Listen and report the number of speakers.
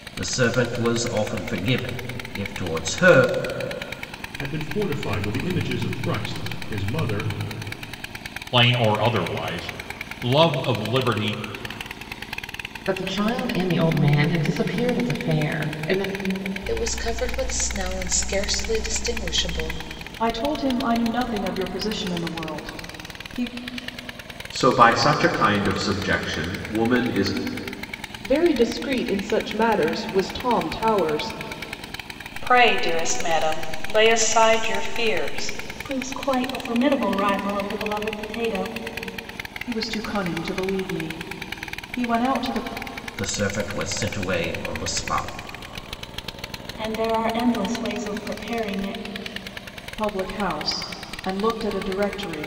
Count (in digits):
10